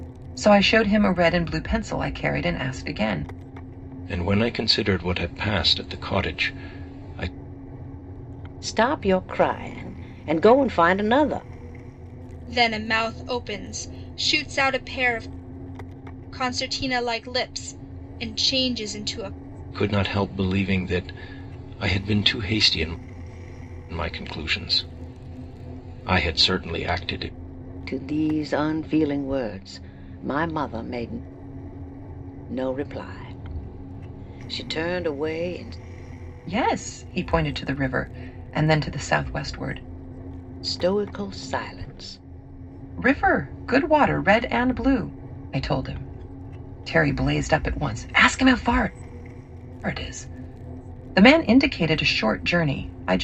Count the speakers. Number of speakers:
4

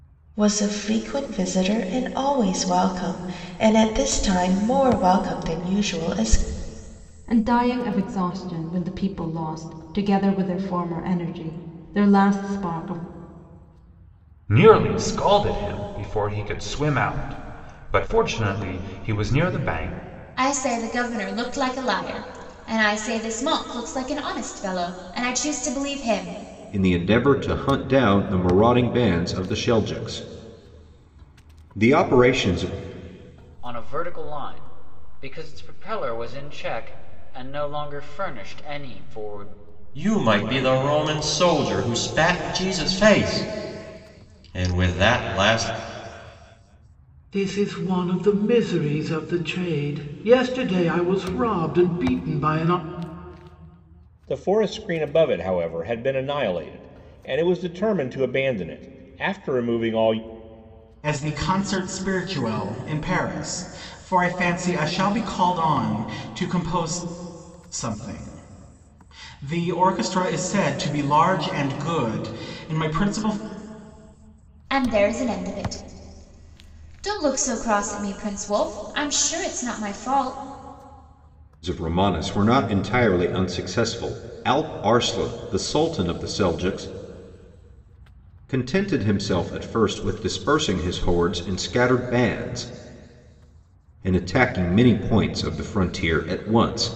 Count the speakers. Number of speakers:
10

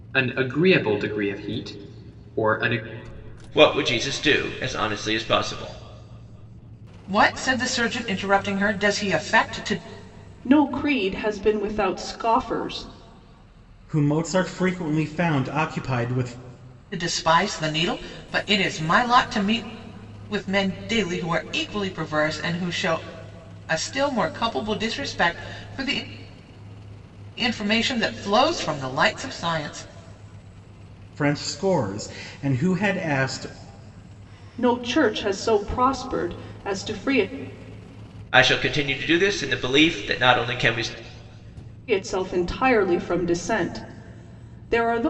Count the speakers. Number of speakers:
5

